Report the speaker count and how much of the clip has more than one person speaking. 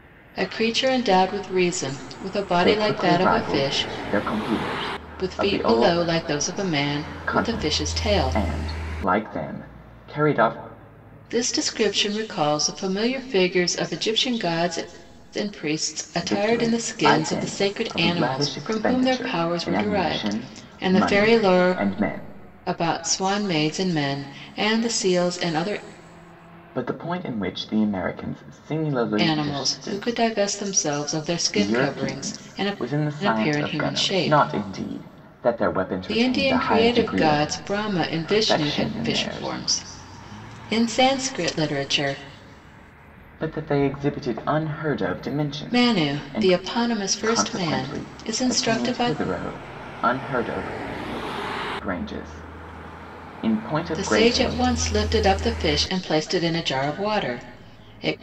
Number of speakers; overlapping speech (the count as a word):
two, about 33%